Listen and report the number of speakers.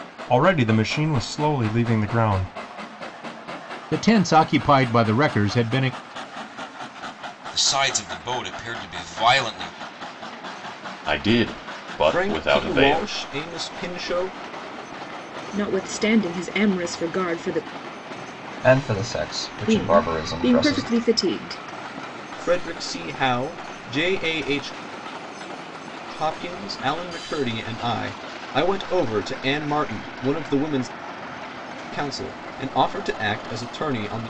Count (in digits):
7